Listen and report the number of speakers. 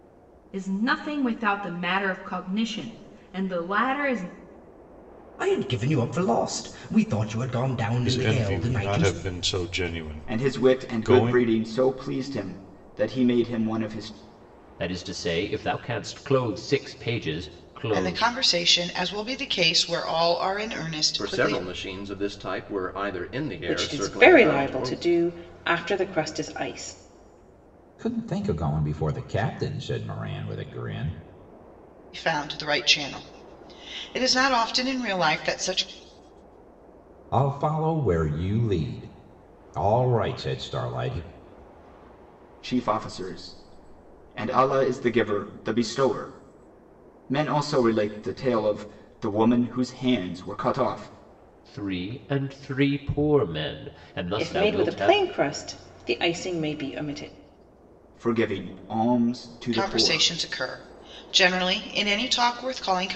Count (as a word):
nine